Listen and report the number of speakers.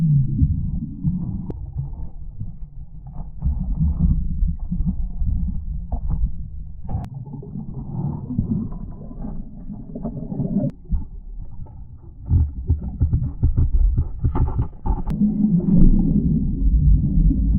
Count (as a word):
zero